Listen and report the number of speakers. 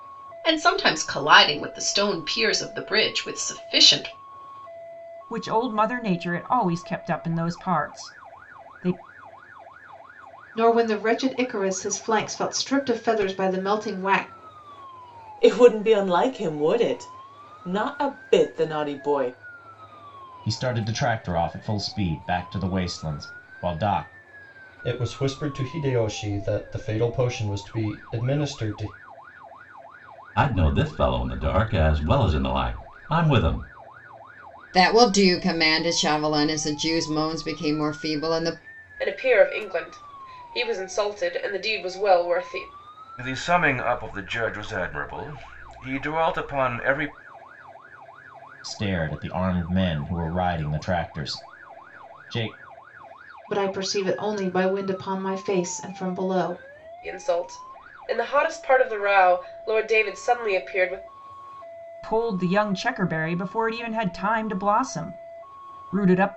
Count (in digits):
10